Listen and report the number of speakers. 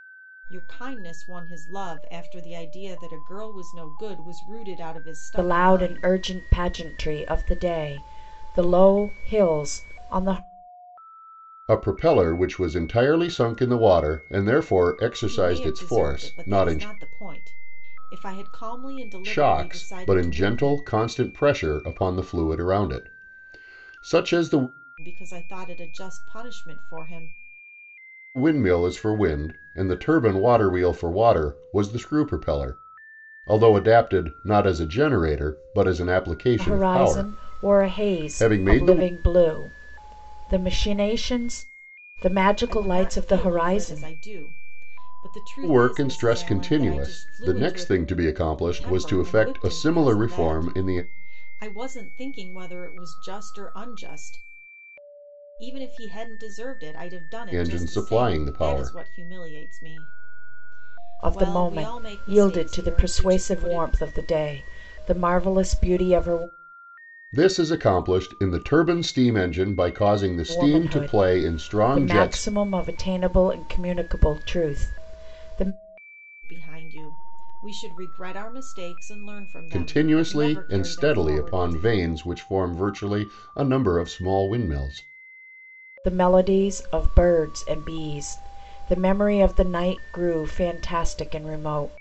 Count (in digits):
3